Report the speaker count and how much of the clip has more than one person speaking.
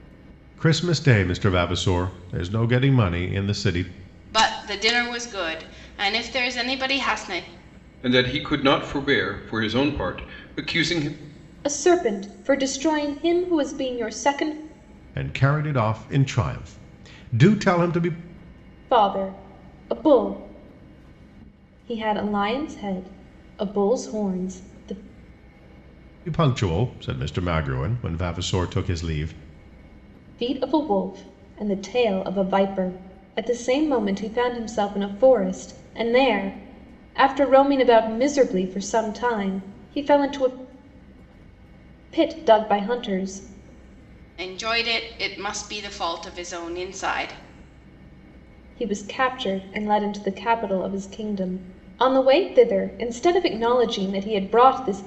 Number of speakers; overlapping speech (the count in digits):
4, no overlap